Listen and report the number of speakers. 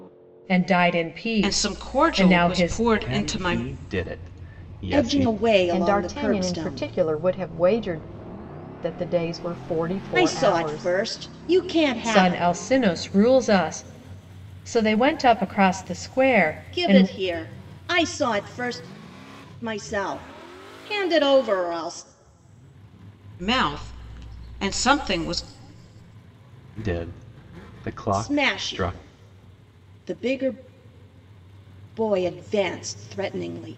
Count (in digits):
5